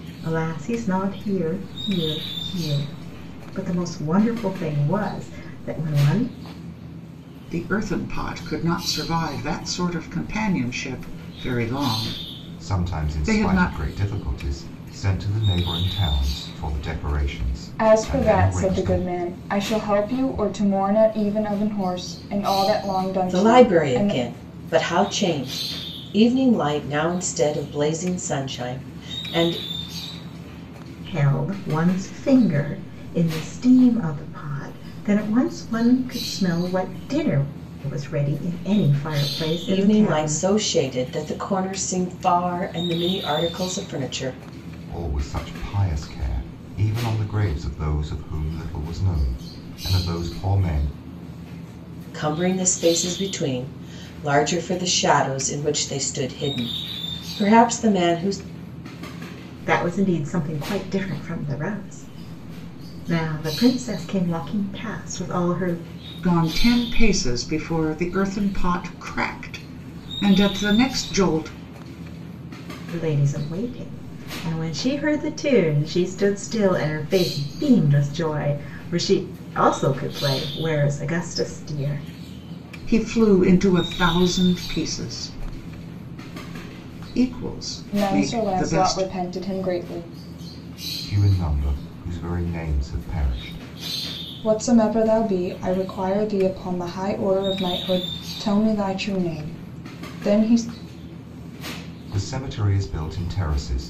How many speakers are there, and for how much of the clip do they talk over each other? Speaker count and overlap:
five, about 5%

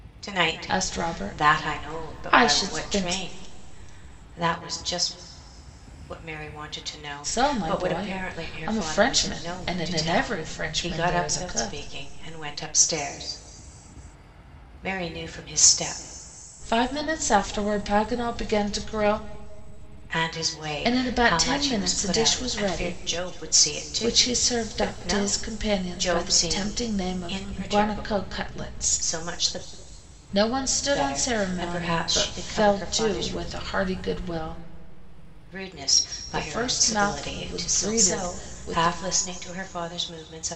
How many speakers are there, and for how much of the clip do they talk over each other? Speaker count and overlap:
two, about 46%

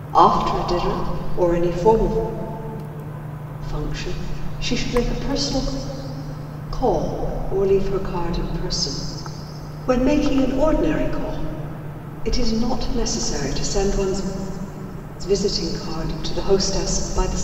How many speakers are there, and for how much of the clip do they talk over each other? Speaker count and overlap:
one, no overlap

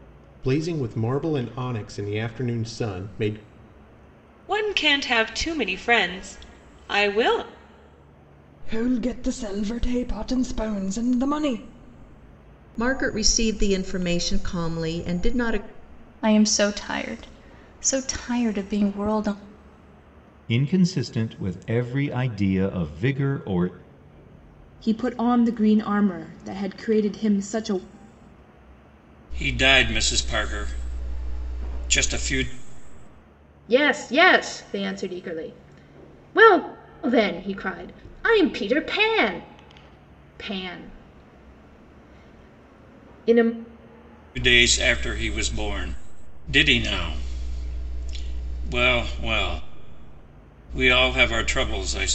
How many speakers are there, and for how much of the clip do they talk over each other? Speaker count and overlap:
nine, no overlap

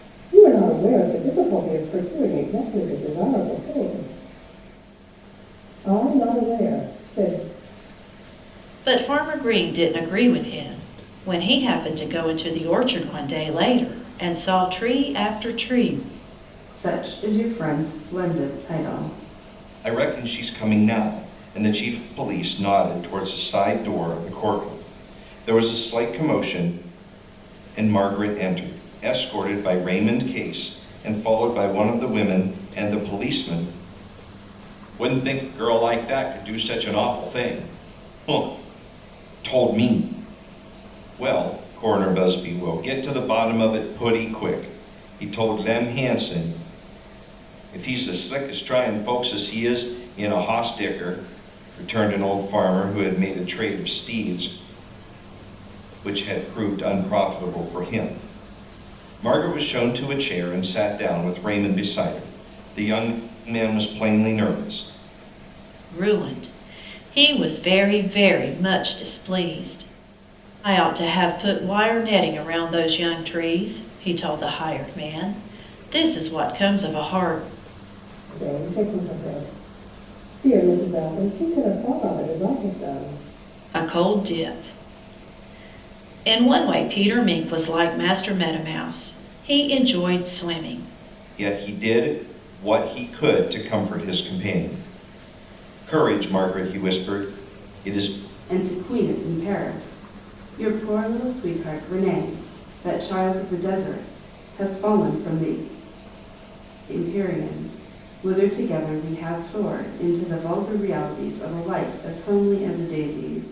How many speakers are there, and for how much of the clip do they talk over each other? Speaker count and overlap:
four, no overlap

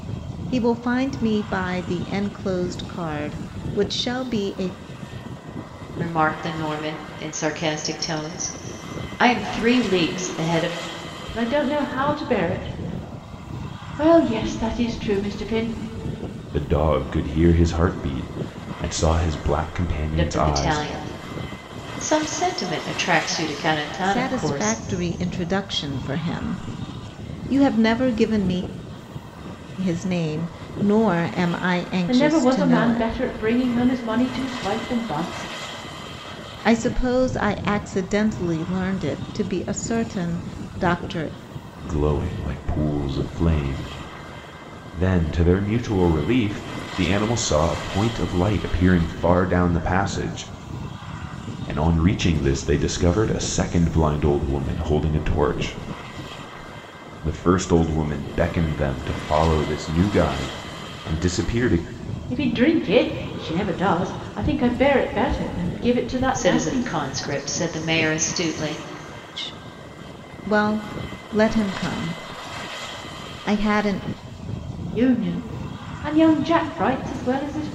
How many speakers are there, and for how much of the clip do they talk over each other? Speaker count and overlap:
four, about 4%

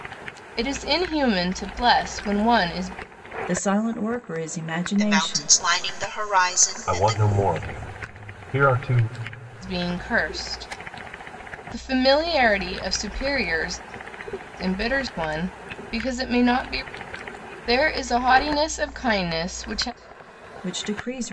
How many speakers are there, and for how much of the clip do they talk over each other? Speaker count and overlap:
four, about 5%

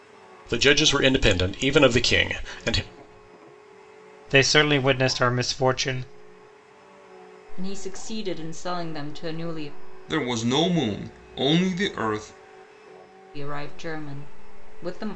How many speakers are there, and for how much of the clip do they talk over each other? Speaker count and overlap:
four, no overlap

